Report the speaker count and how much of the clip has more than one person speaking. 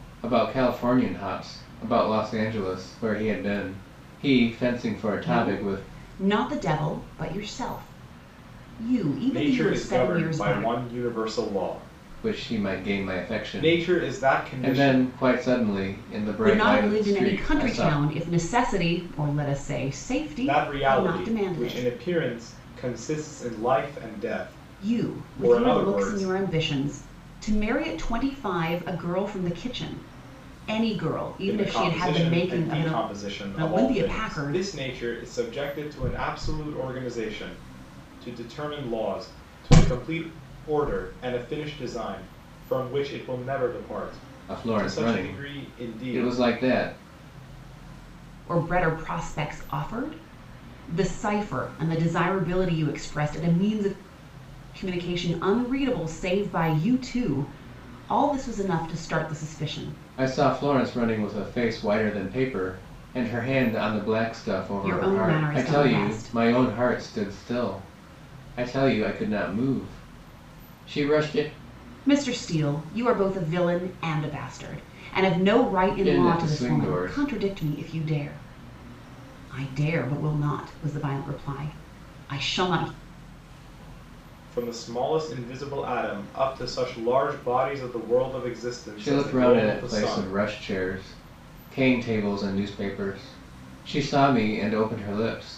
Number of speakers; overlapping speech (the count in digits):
3, about 19%